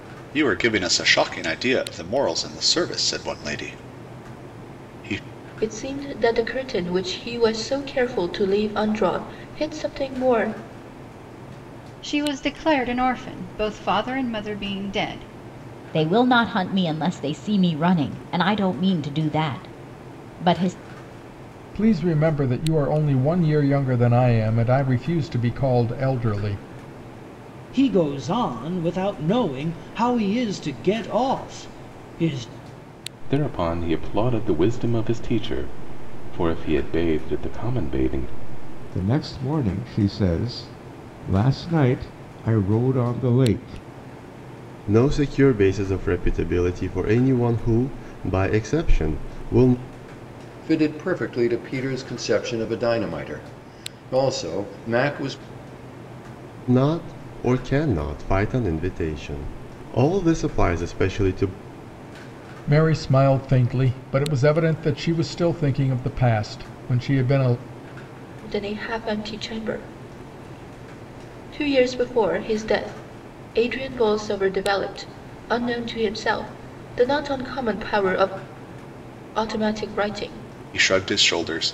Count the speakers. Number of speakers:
10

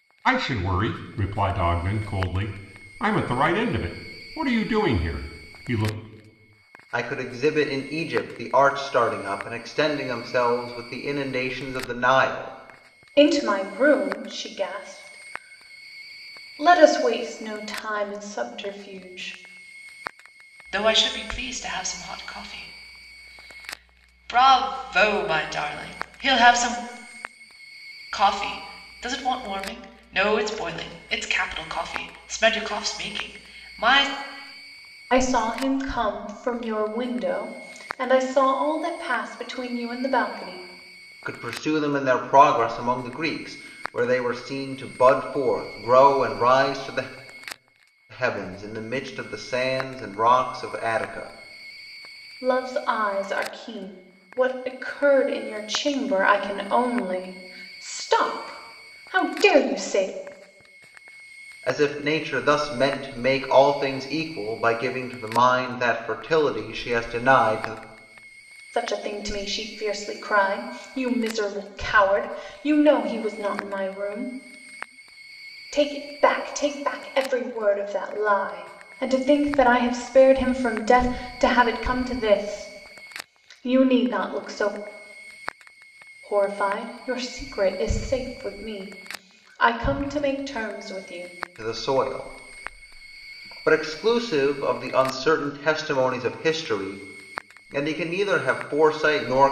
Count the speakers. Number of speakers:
4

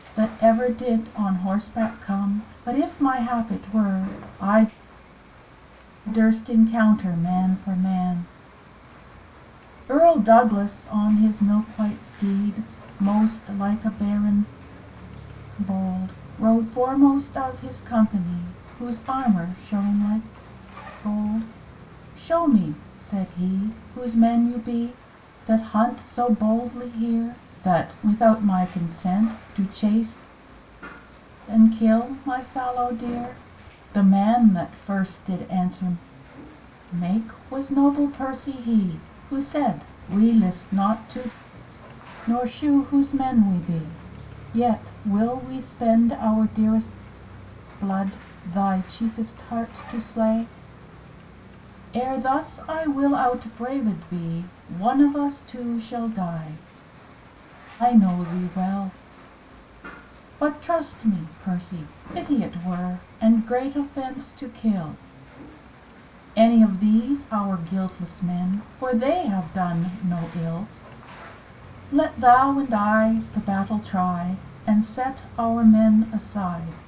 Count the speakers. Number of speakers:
1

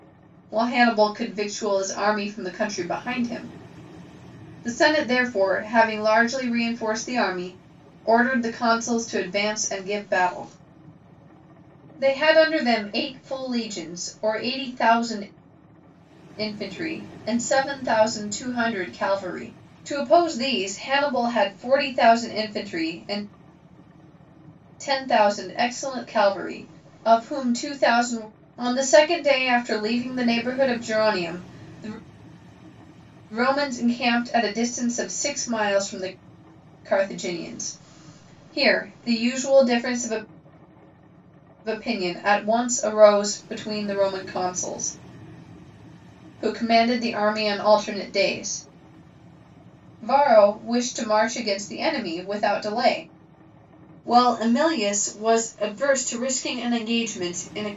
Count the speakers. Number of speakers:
1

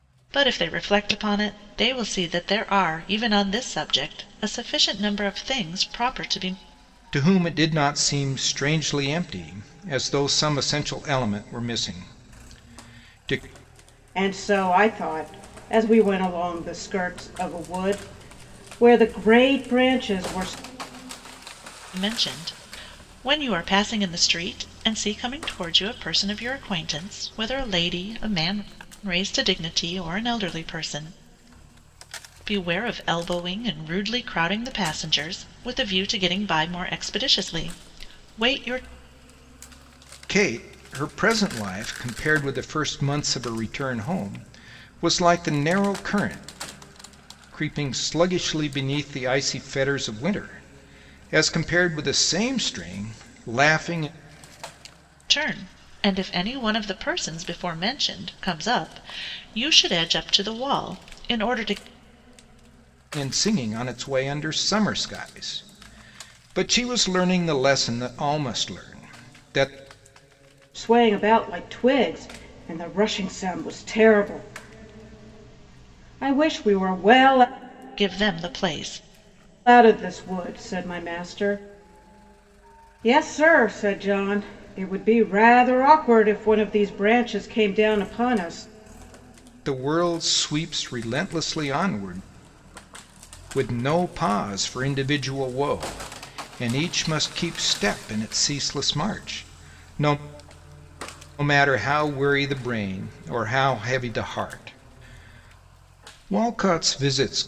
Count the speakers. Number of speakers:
3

